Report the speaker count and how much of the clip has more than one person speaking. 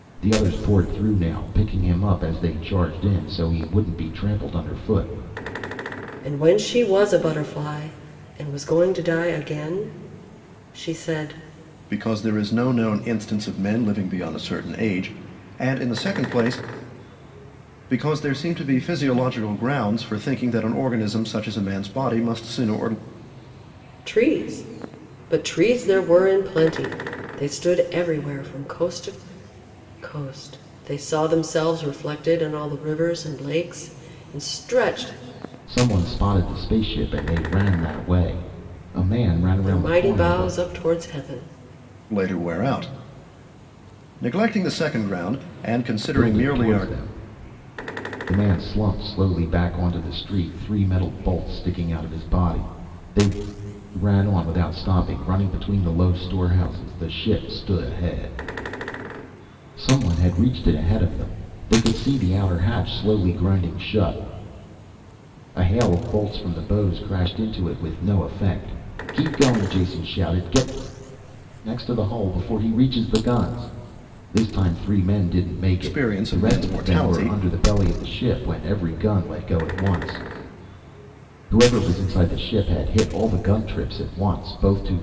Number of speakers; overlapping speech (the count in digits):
3, about 4%